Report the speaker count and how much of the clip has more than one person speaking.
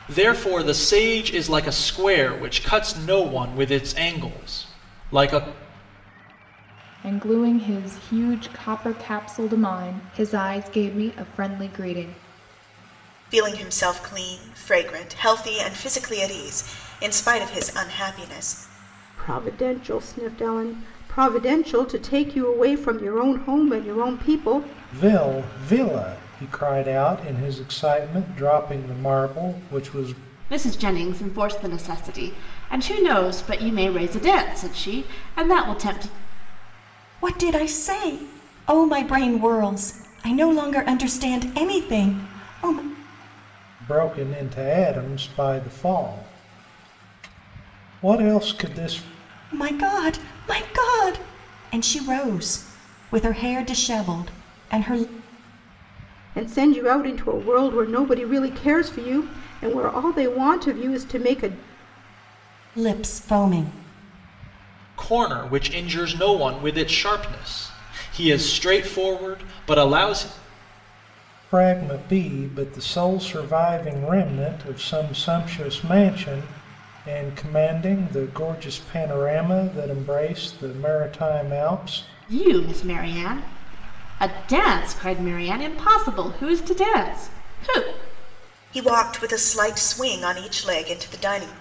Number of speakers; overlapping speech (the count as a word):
seven, no overlap